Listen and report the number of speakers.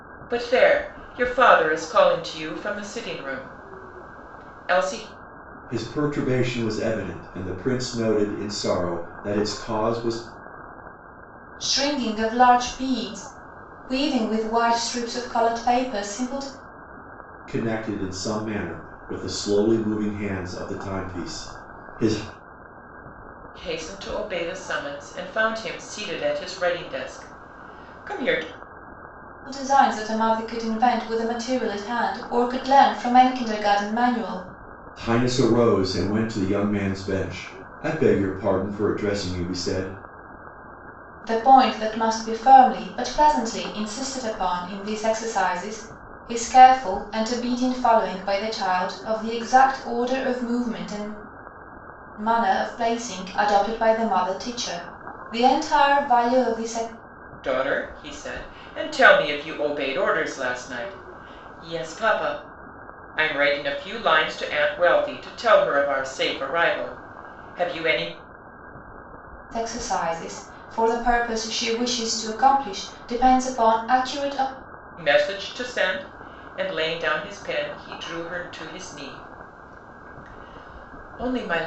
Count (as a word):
three